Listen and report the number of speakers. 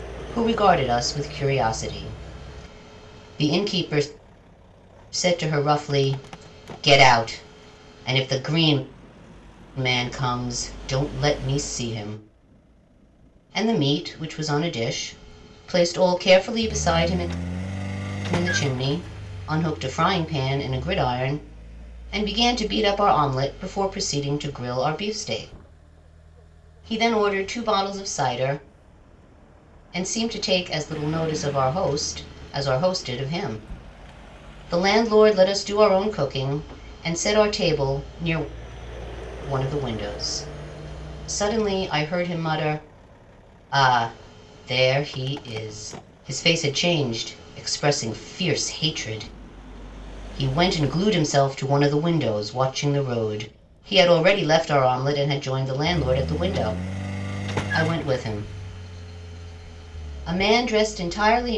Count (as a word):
one